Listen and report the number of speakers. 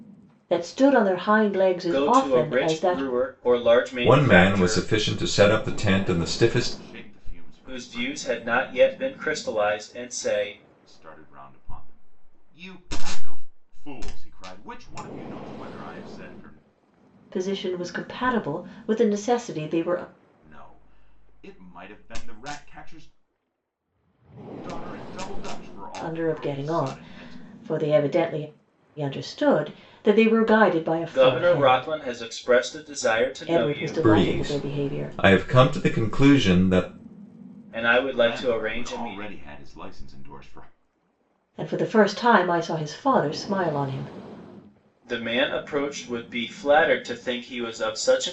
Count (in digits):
4